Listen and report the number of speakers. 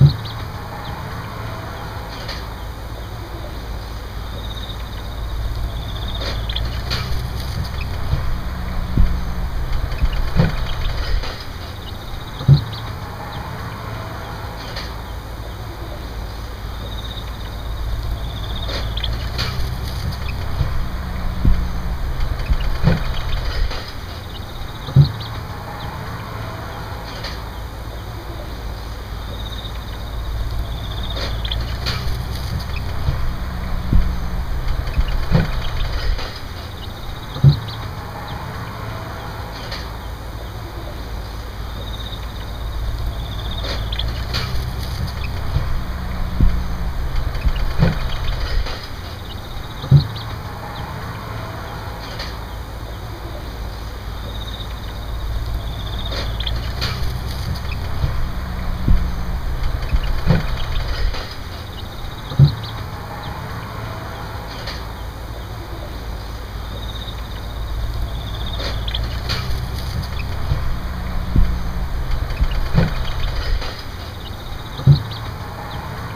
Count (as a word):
zero